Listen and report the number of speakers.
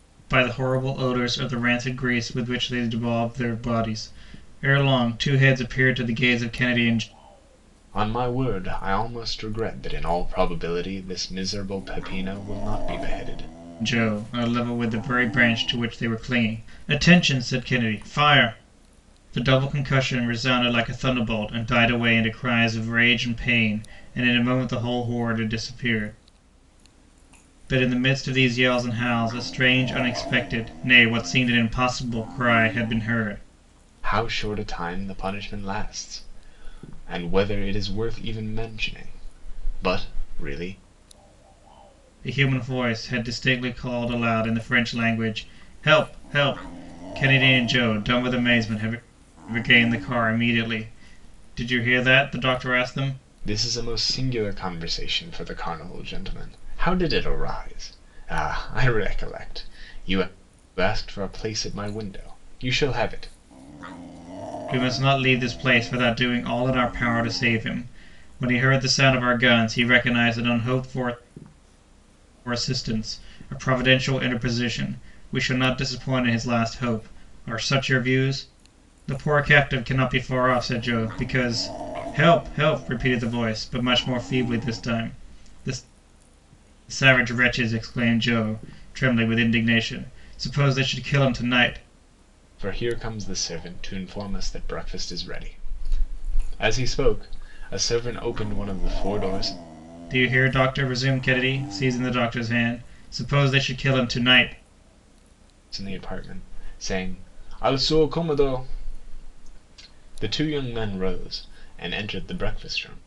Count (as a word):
two